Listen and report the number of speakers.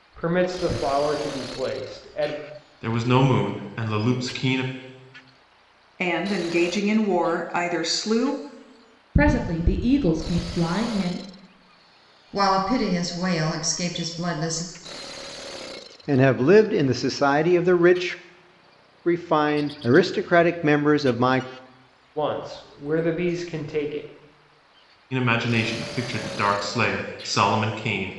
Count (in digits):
6